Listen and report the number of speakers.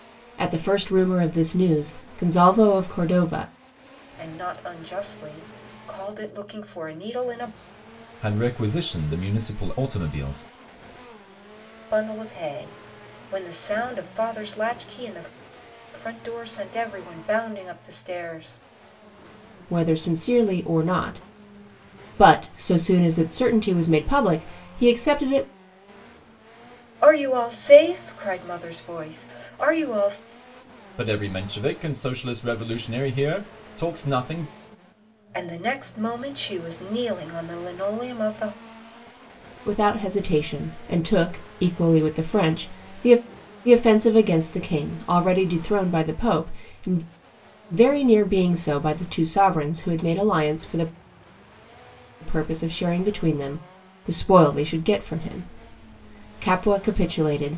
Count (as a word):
three